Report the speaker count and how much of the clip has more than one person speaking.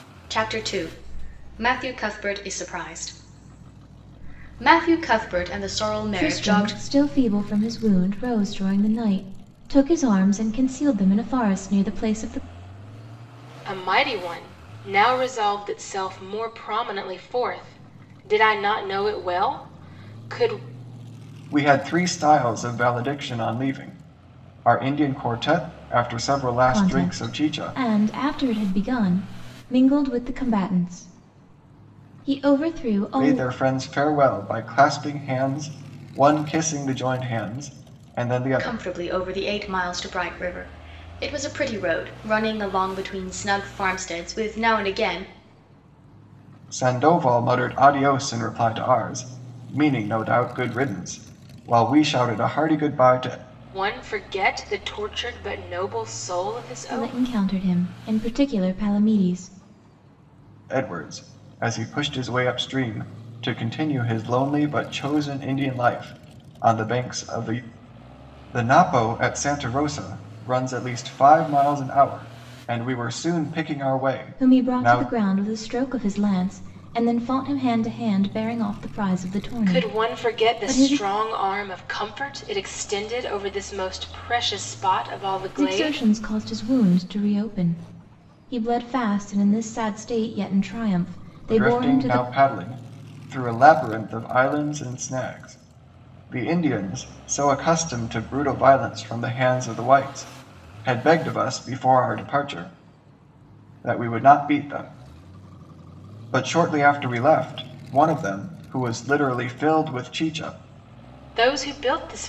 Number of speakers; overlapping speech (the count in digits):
4, about 6%